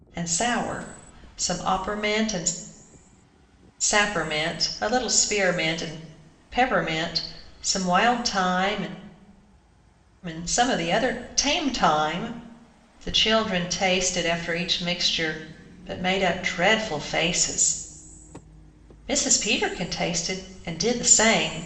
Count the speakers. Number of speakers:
1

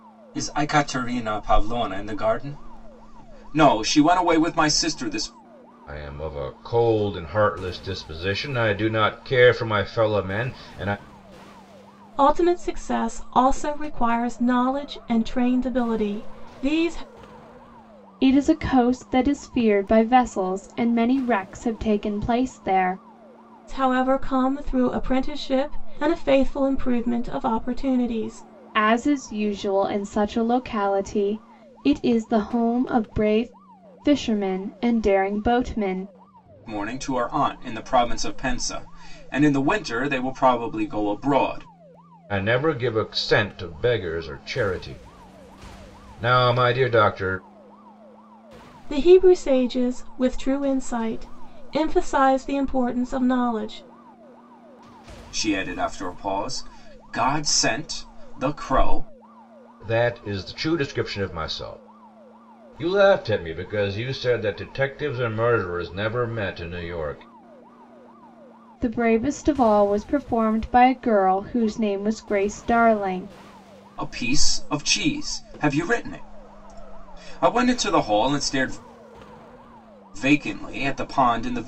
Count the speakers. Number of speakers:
4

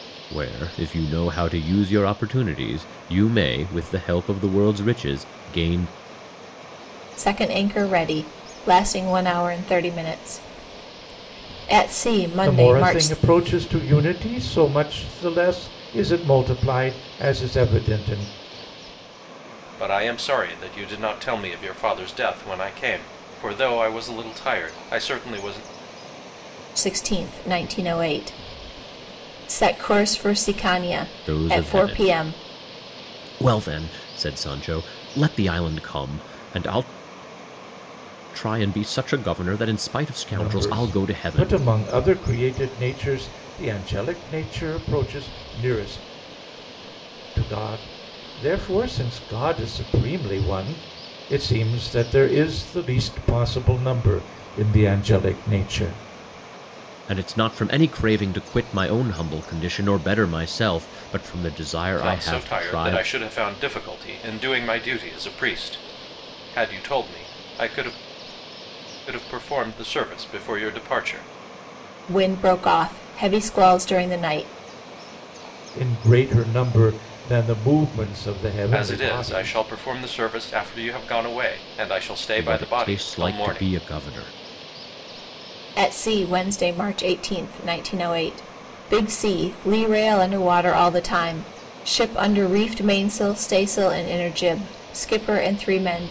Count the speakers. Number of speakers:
4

